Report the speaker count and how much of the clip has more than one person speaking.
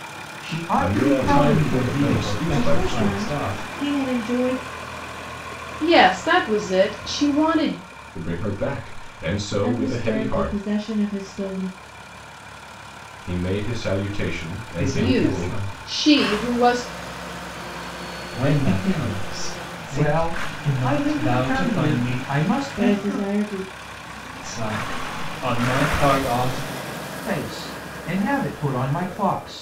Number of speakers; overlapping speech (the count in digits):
5, about 32%